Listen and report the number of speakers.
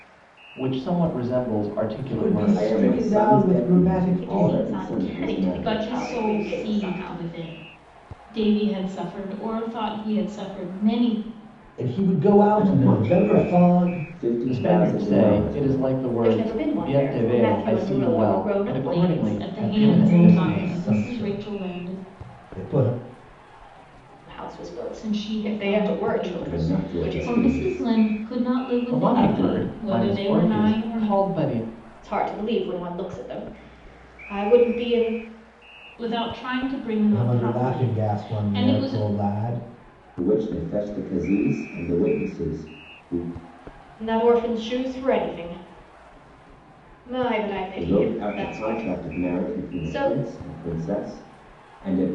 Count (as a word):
five